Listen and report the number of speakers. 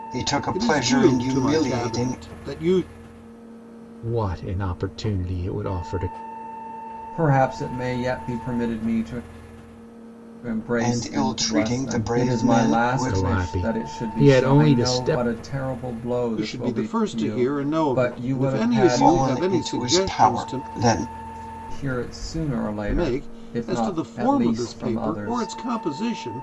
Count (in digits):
4